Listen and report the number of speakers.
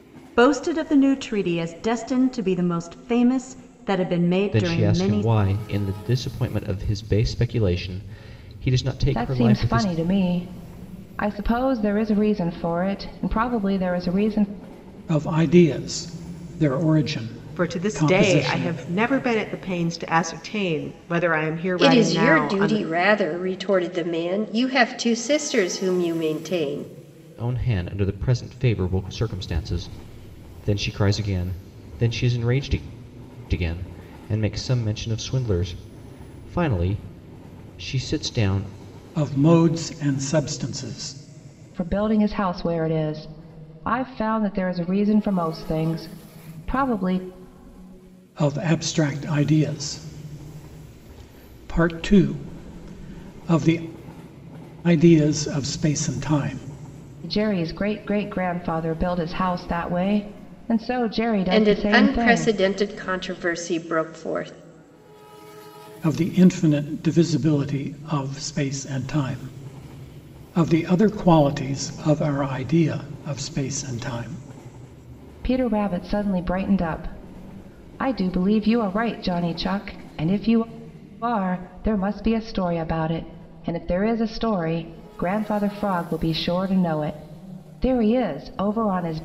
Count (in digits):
6